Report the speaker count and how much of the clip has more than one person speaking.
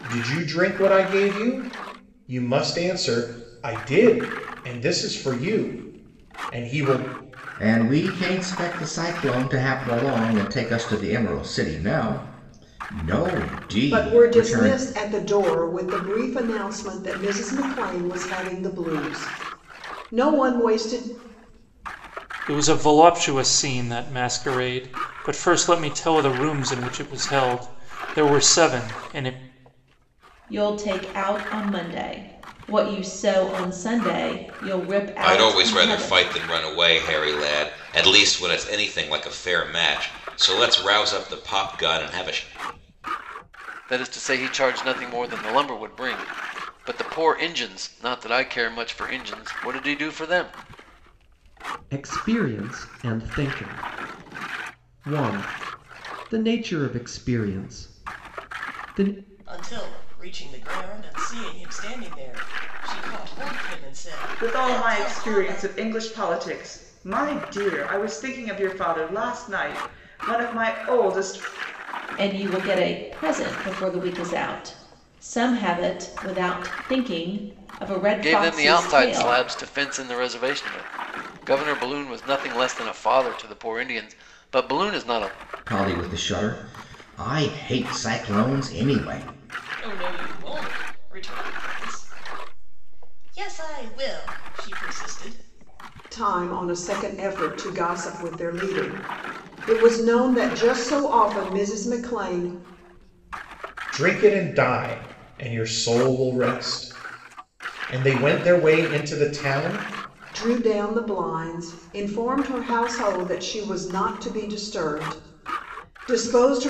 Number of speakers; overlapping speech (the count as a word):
ten, about 4%